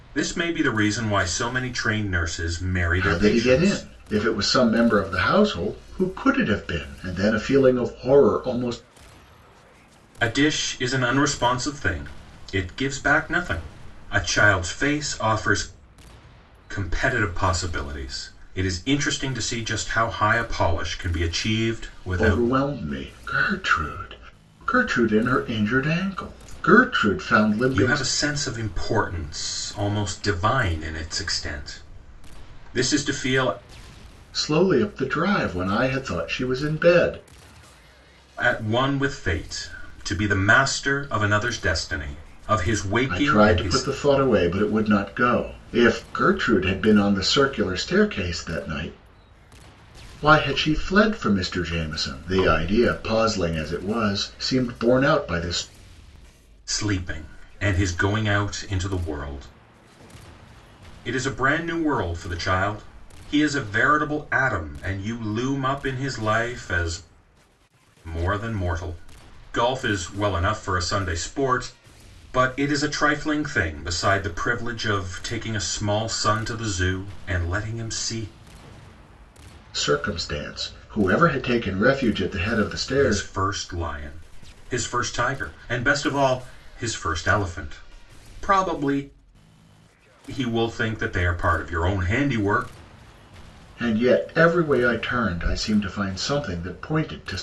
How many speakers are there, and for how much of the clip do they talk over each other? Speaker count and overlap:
two, about 3%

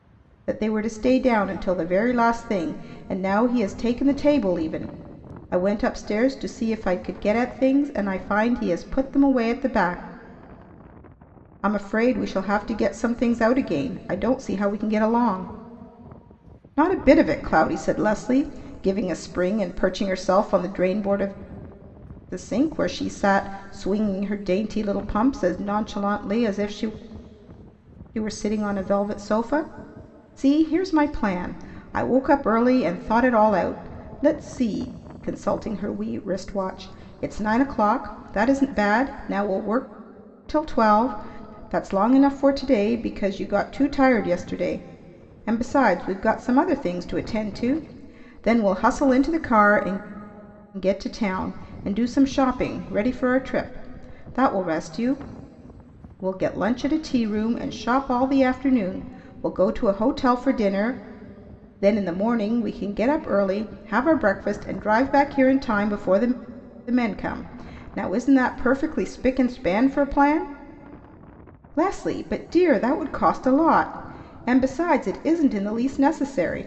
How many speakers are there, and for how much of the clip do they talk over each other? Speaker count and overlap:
one, no overlap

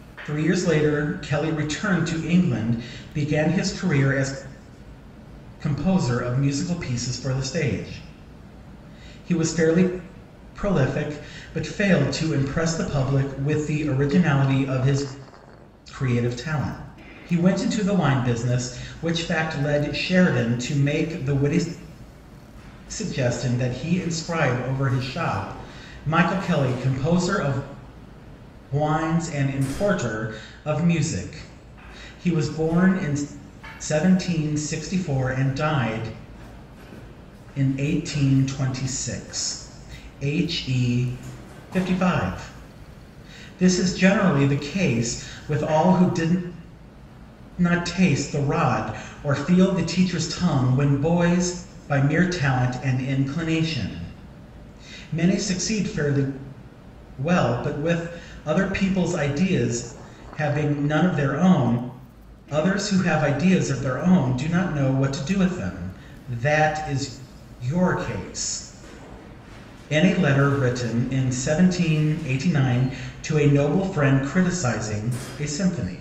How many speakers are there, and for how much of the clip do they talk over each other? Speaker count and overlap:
one, no overlap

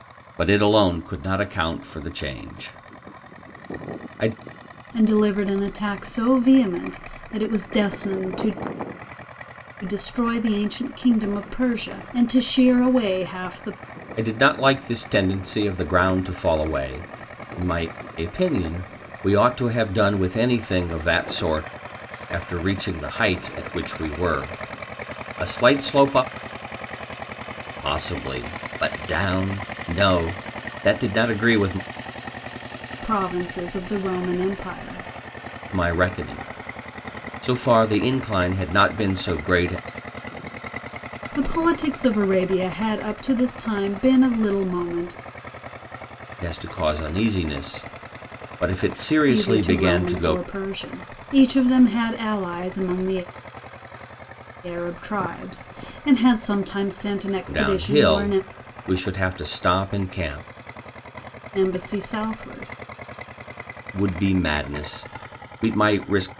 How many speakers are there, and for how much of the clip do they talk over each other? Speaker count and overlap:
two, about 3%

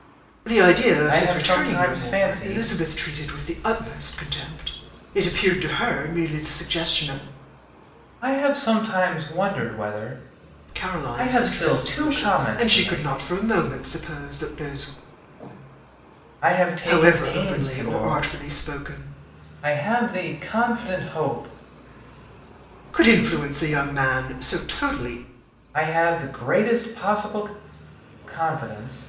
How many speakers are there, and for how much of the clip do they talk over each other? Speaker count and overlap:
two, about 18%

